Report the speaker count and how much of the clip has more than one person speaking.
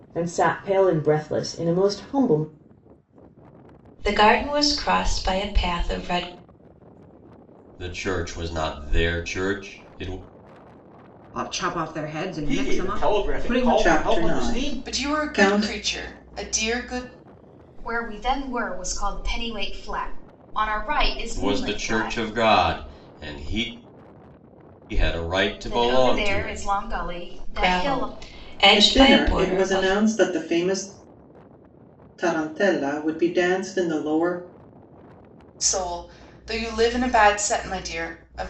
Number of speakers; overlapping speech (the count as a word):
eight, about 19%